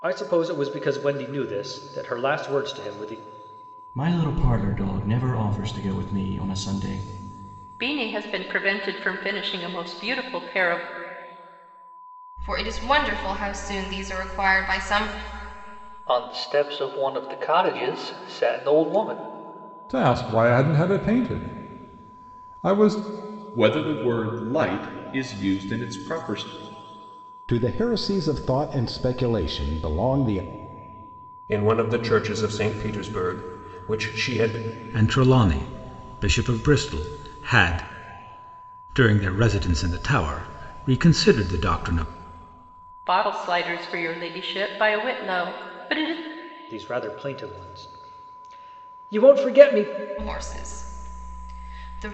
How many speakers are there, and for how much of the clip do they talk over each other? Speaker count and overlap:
10, no overlap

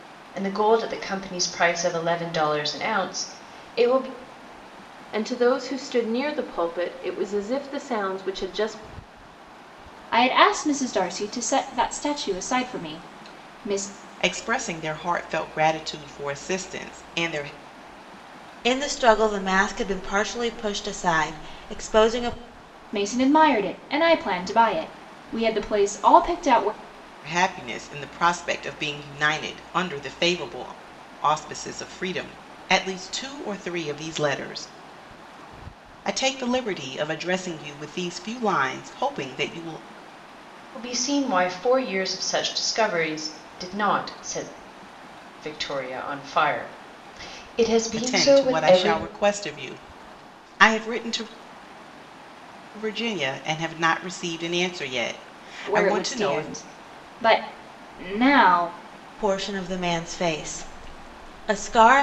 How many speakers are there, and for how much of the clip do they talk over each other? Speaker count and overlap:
5, about 3%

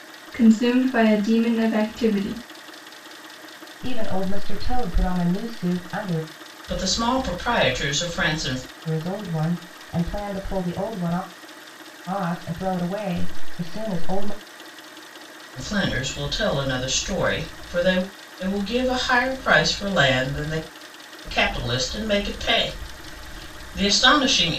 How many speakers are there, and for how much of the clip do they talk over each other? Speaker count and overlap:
3, no overlap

